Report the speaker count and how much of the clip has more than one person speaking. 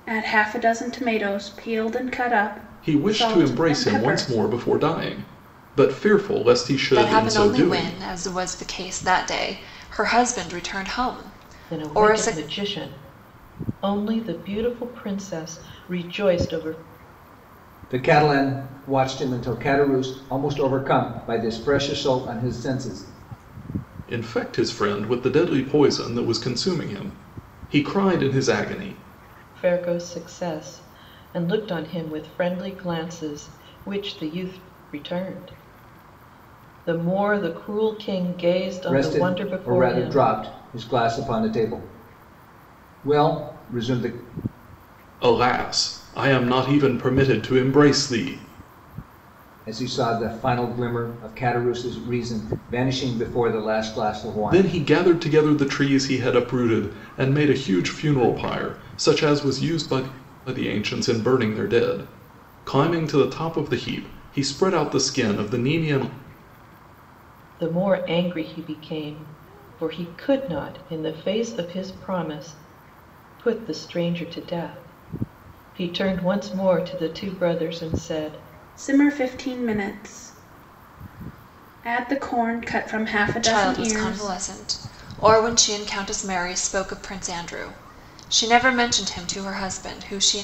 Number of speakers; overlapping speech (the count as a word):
five, about 7%